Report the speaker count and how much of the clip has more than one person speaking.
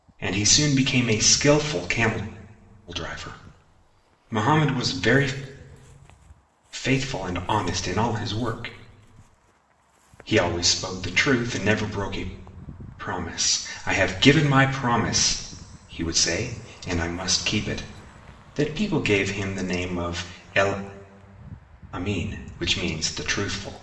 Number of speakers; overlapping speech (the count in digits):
1, no overlap